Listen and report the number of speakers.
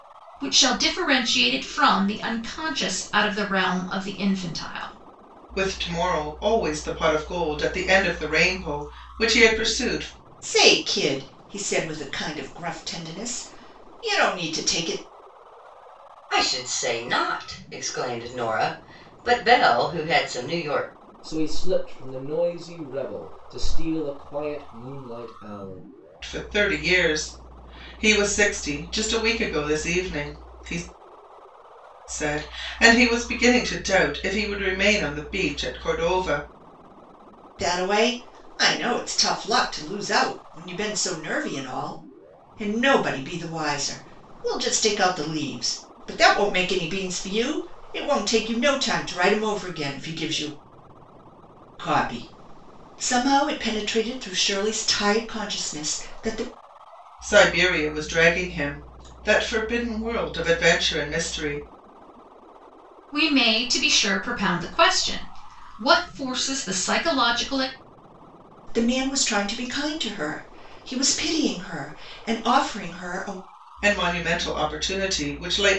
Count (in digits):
5